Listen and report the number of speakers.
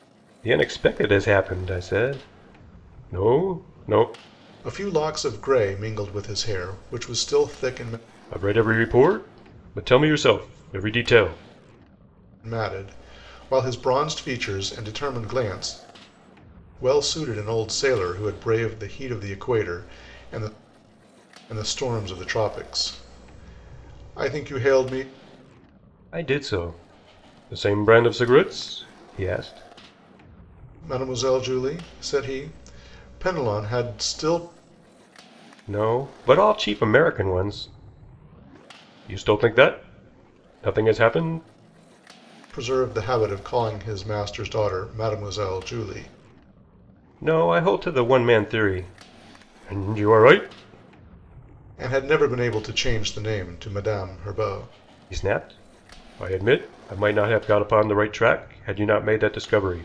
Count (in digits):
2